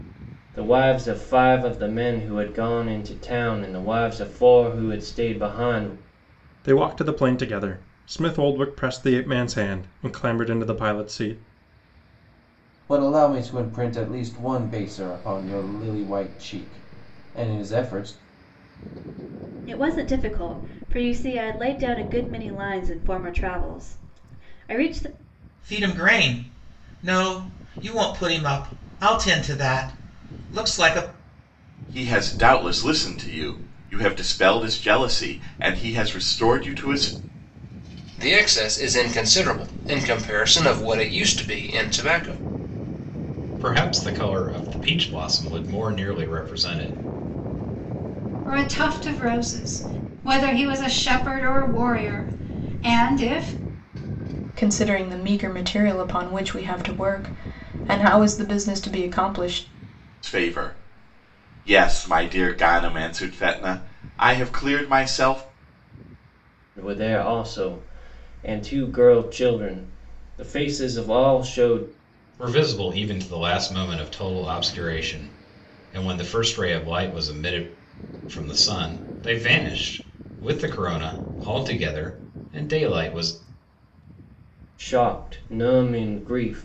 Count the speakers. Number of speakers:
ten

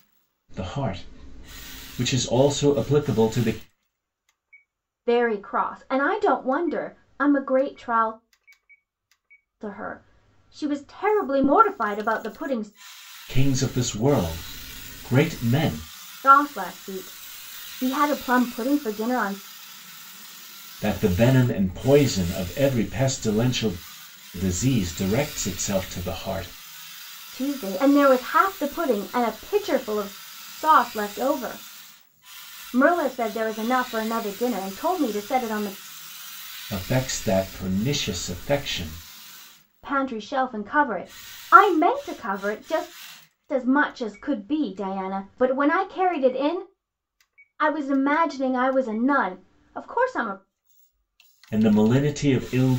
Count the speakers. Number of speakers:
two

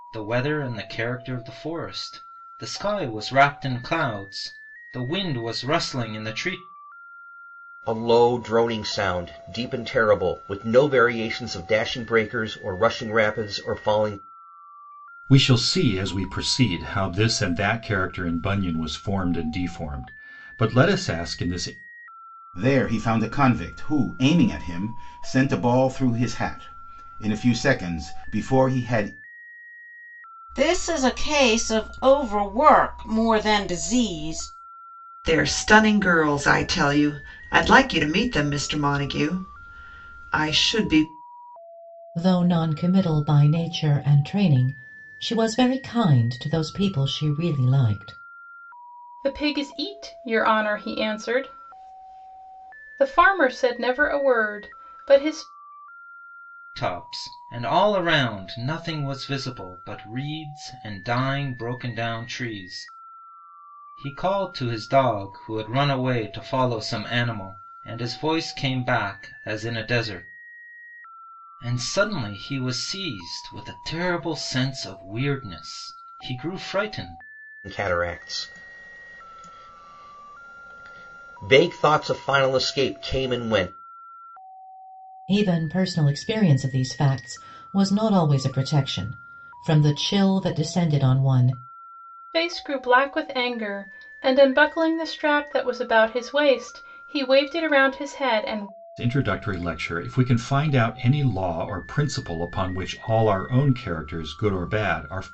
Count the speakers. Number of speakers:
eight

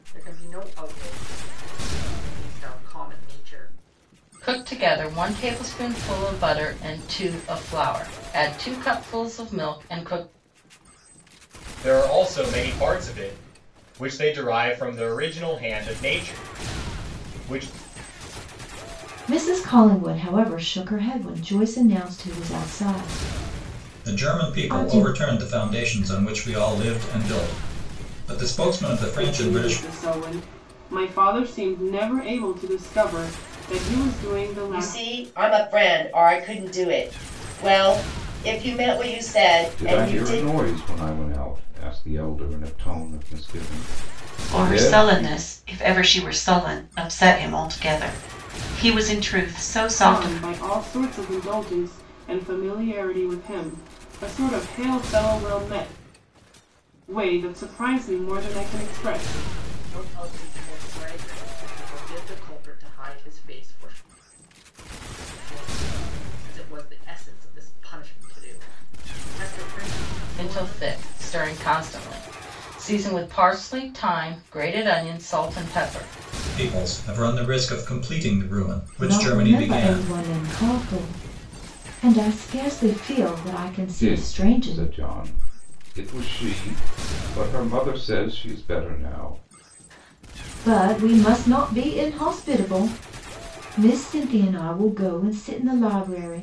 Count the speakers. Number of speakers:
nine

